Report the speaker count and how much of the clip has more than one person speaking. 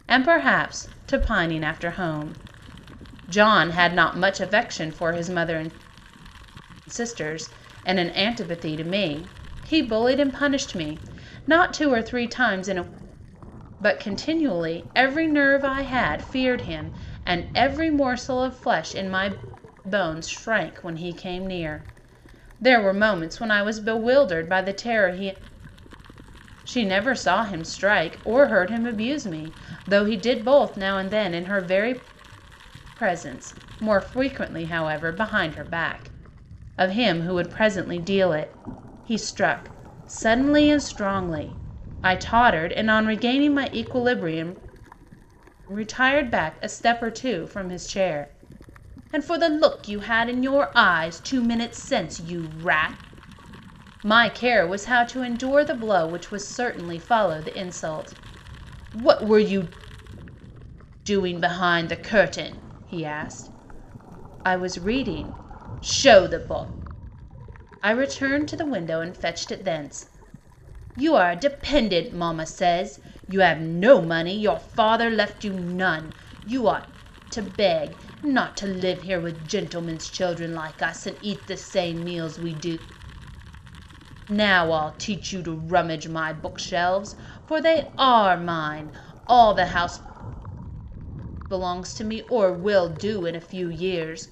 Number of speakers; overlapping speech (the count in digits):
1, no overlap